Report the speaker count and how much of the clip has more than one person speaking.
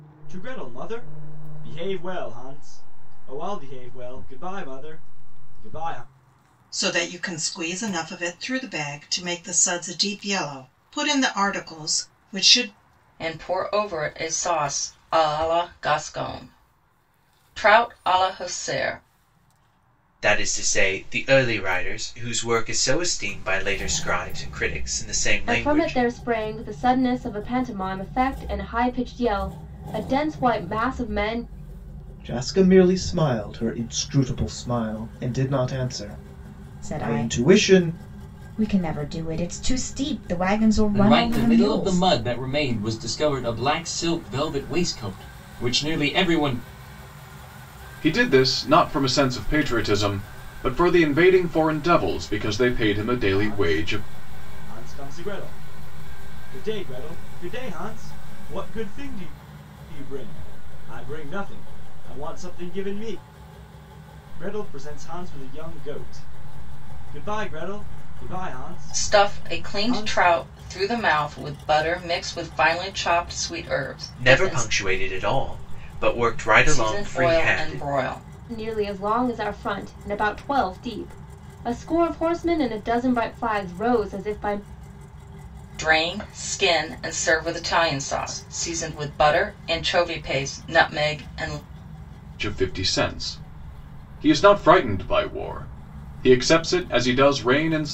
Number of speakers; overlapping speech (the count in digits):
9, about 7%